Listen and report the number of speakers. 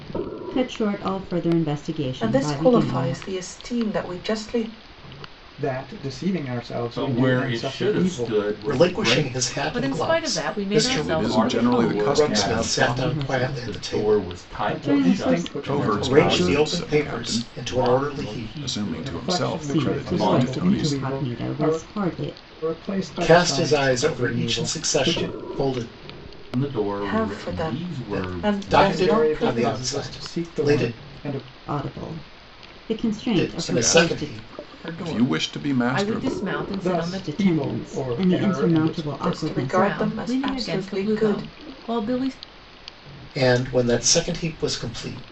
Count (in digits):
7